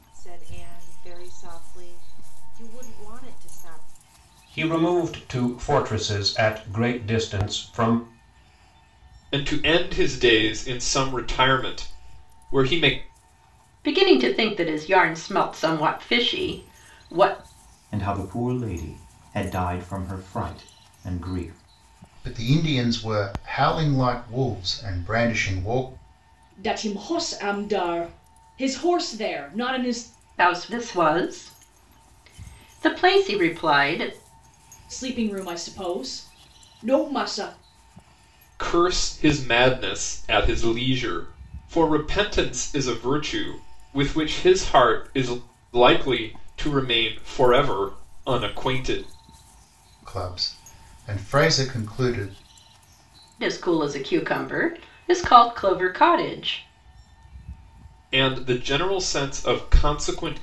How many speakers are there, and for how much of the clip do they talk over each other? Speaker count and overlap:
seven, no overlap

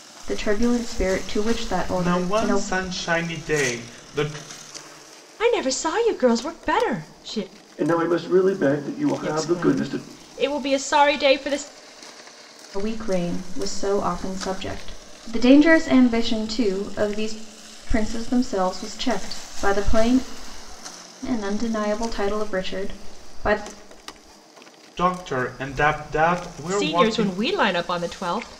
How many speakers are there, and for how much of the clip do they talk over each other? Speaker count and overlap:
four, about 8%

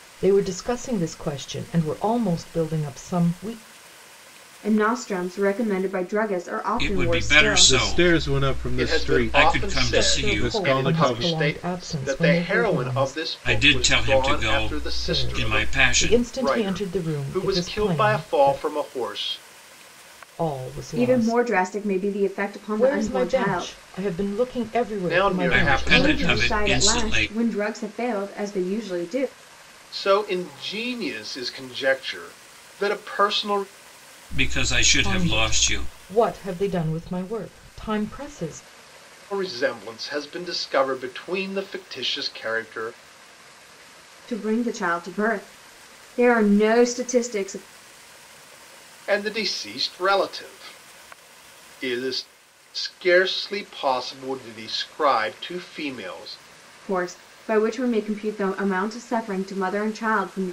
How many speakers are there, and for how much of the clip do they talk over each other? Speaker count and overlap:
five, about 27%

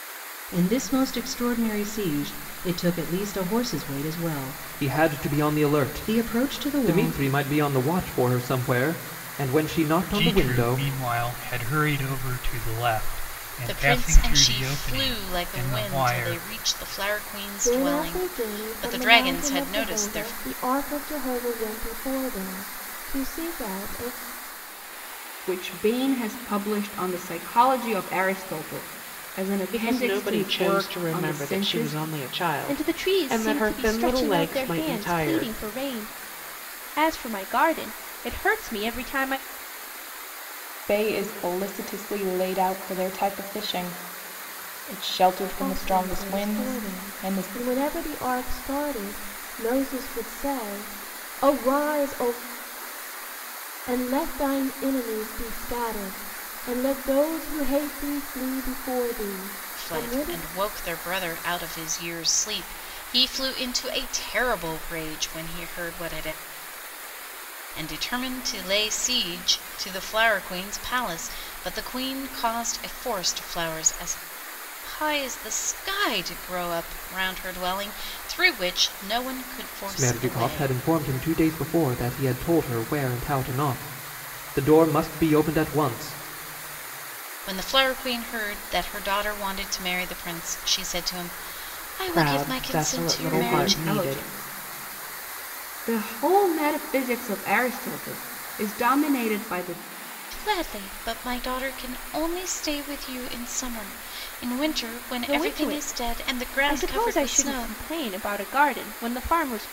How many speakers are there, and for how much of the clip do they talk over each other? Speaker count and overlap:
nine, about 21%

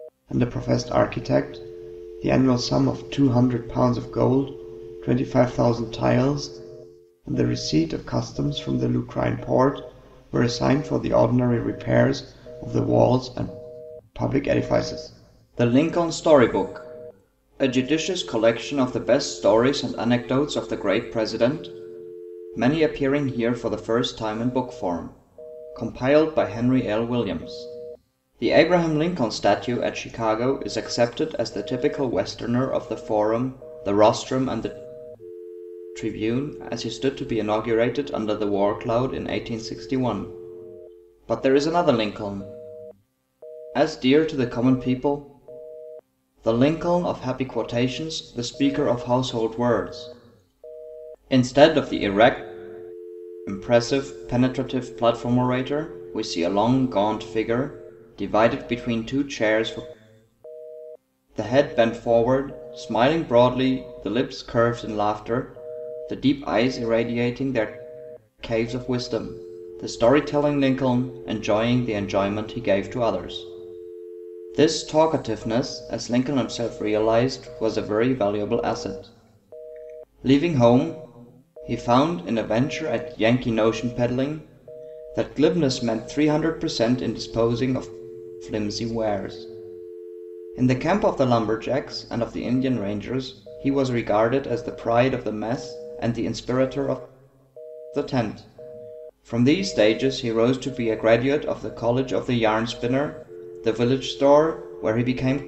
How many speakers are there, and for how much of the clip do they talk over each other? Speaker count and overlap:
one, no overlap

